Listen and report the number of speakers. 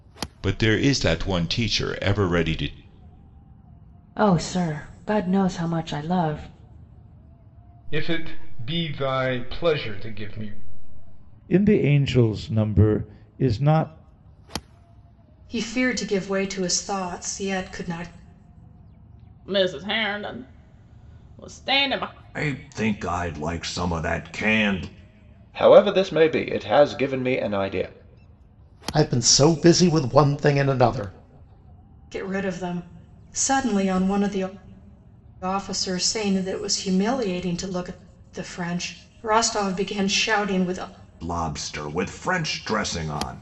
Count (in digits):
9